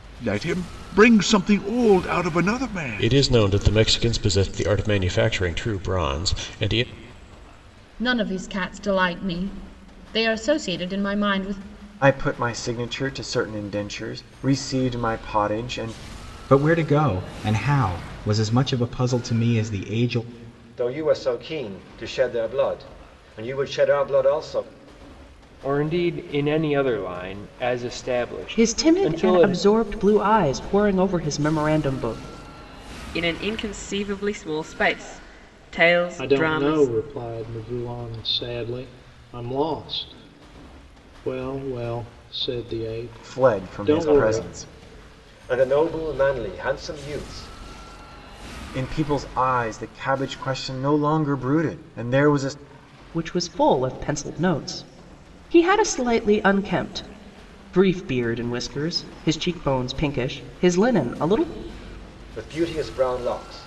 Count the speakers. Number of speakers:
10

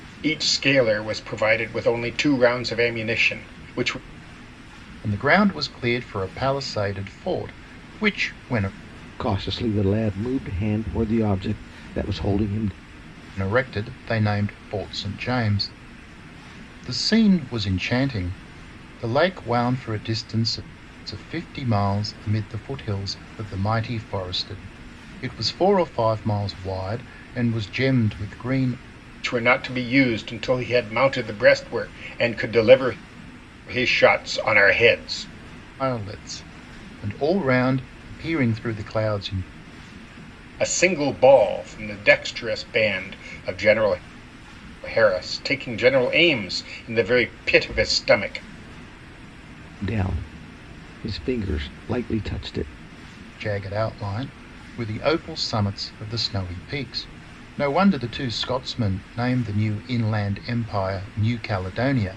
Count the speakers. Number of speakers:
3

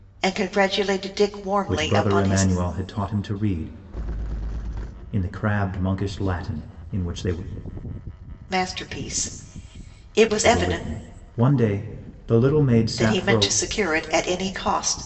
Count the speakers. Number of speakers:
2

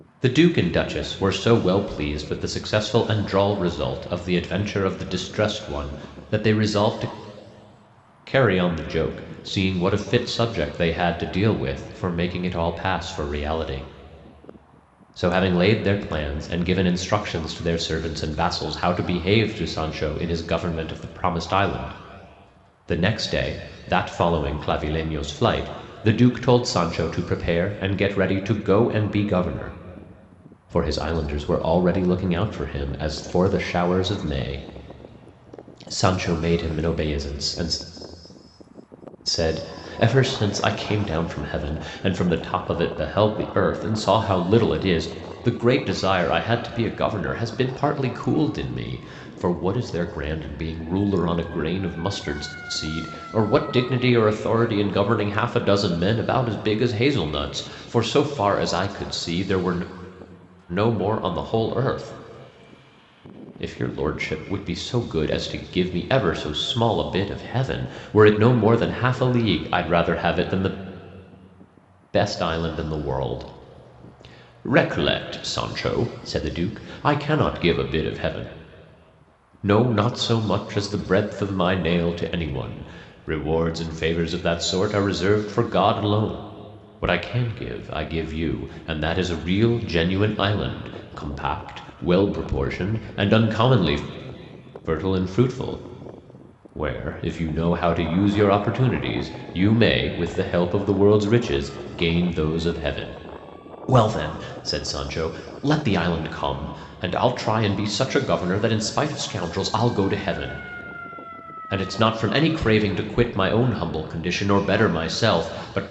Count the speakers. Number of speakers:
1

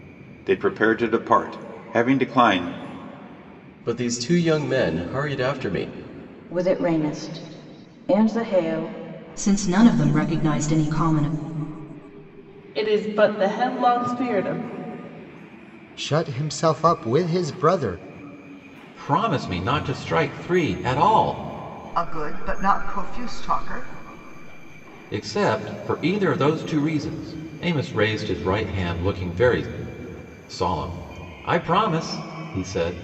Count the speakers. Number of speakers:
8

